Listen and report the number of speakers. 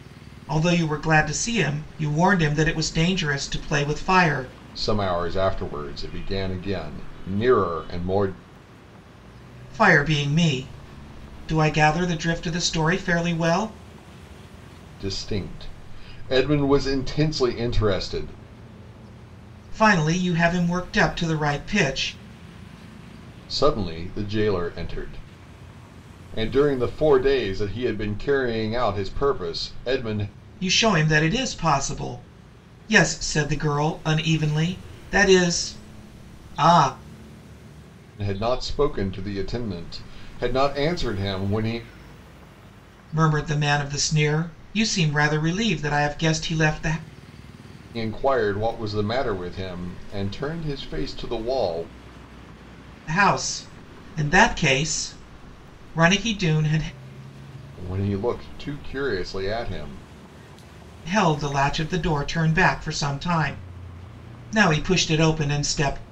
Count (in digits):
2